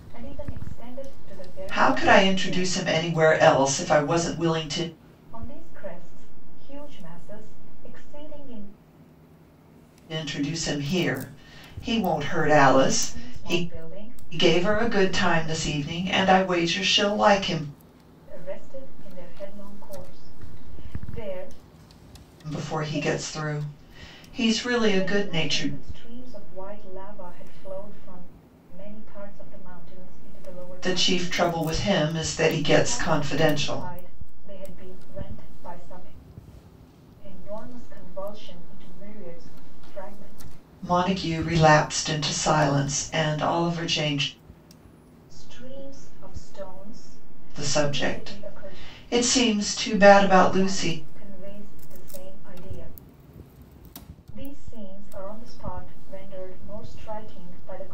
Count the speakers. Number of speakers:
two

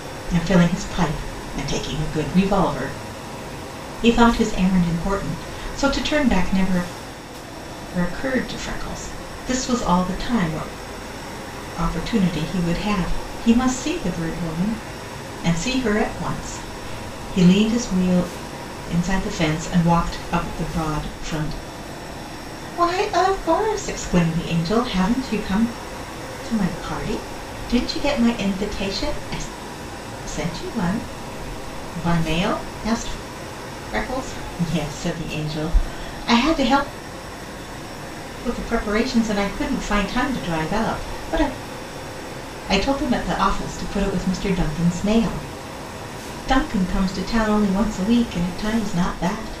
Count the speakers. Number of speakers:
one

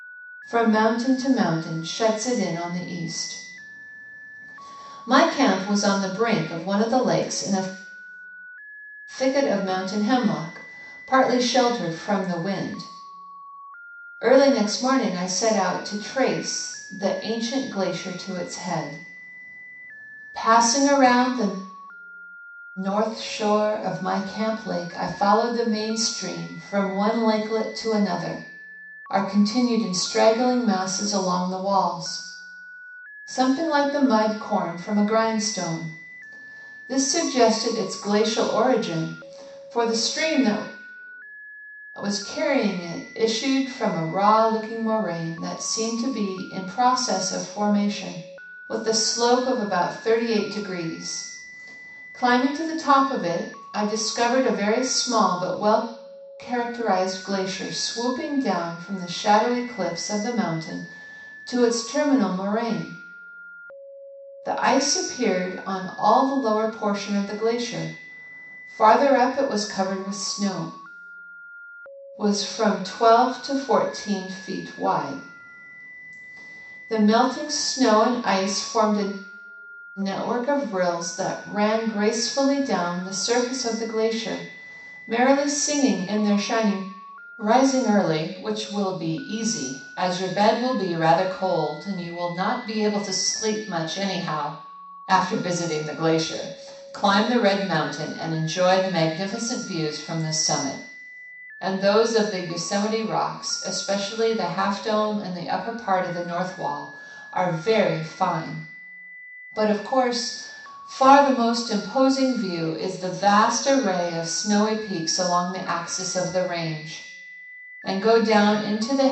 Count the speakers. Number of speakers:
one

